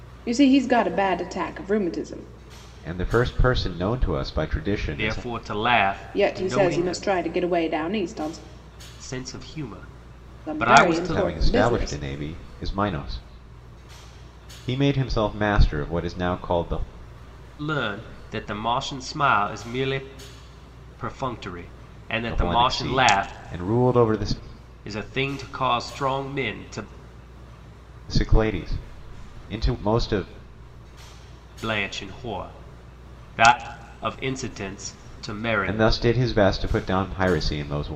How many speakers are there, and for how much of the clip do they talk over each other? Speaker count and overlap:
three, about 12%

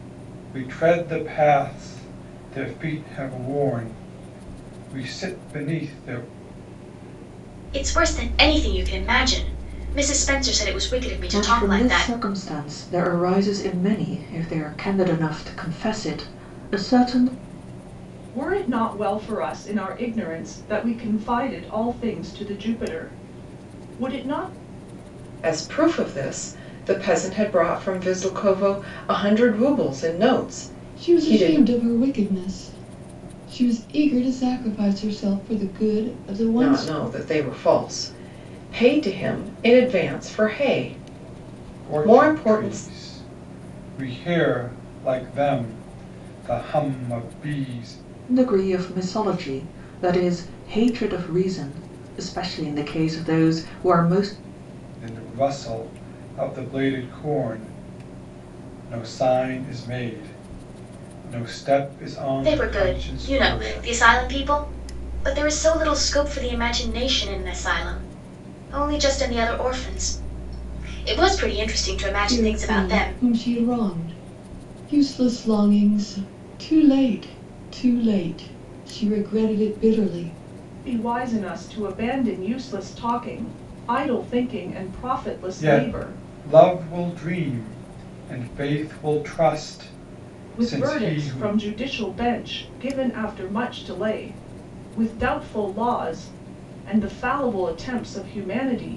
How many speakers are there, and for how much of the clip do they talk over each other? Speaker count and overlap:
six, about 7%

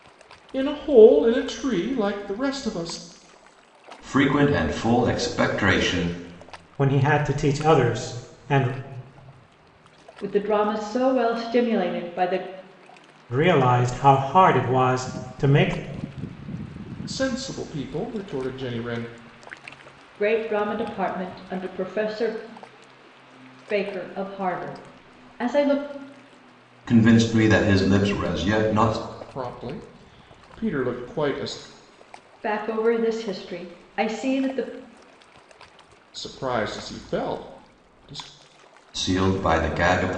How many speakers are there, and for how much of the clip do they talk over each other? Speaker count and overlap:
four, no overlap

